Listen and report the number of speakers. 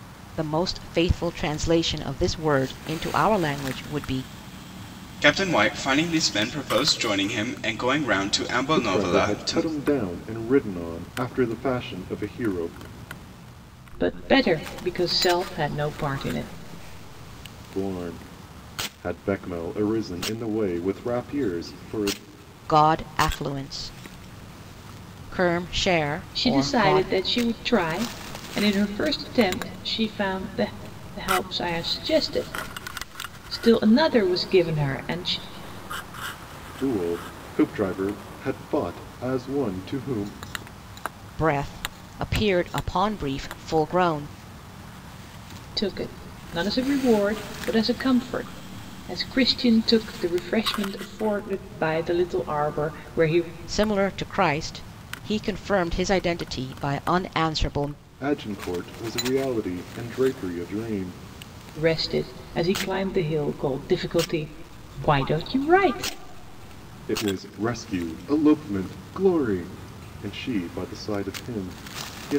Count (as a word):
four